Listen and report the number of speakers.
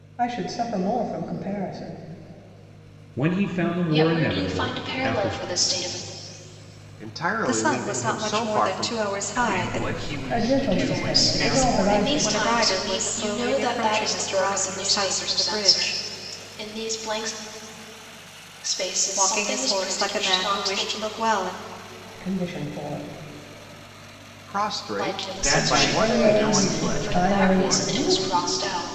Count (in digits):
7